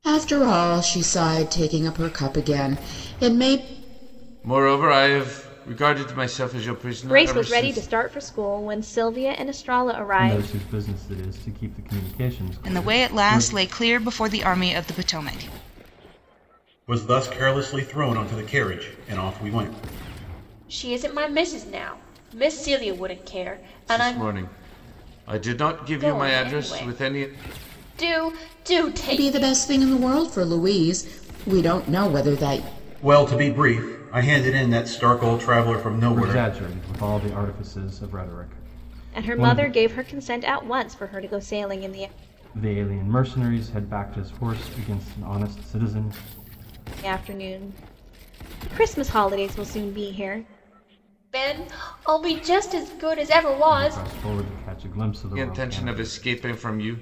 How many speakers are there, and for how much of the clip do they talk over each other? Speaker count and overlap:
seven, about 11%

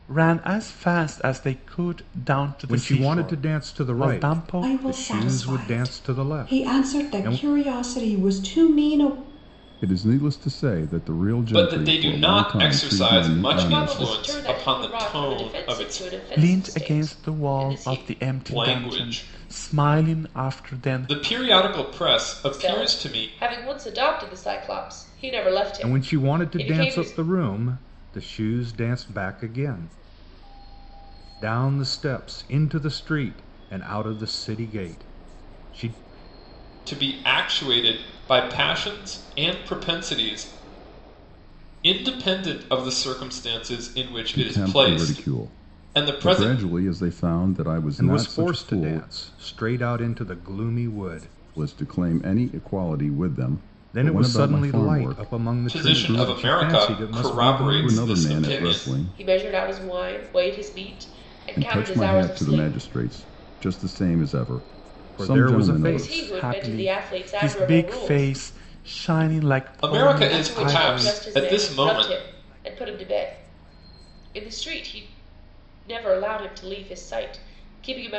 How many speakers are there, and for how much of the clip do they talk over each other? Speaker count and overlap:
six, about 40%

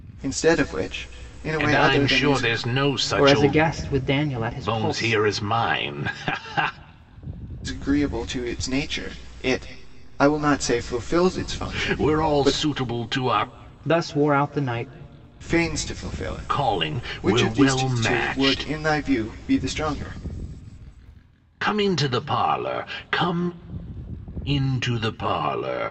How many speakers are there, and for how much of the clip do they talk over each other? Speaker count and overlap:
three, about 20%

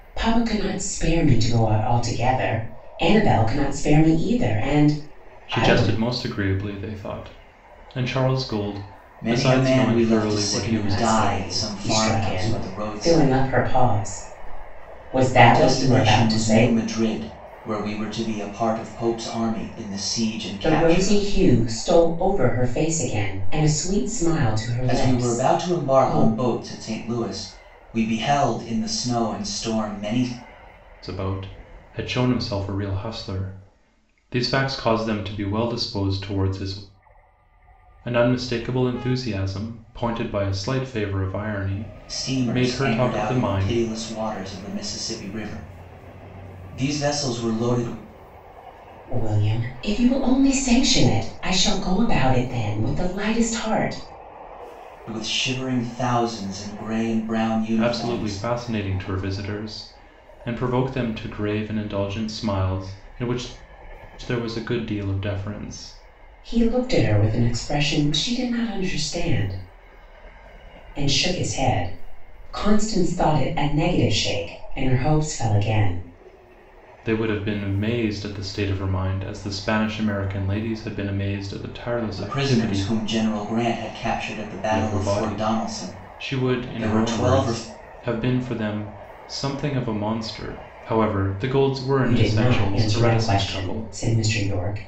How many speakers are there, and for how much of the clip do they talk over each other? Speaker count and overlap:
three, about 17%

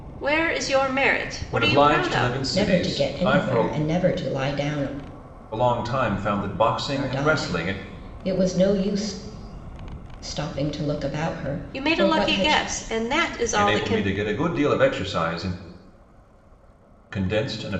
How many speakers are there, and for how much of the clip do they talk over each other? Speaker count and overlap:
three, about 25%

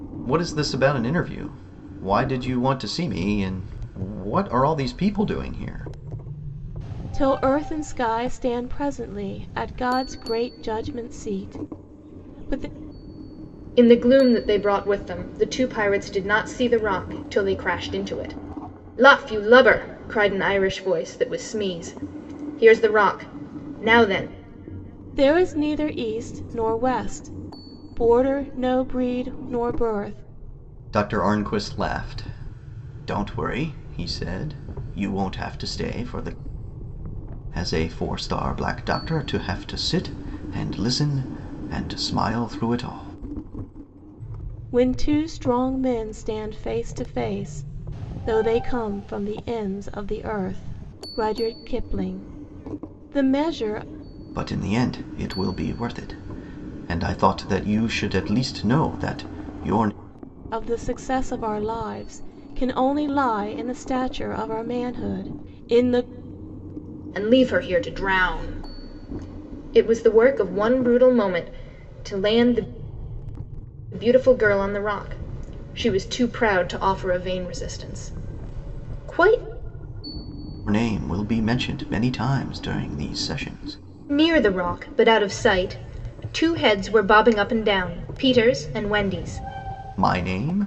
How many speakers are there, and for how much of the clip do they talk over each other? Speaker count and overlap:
three, no overlap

